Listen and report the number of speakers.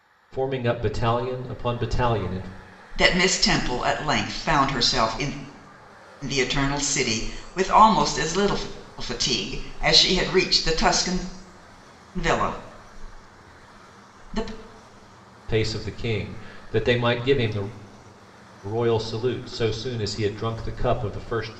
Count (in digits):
2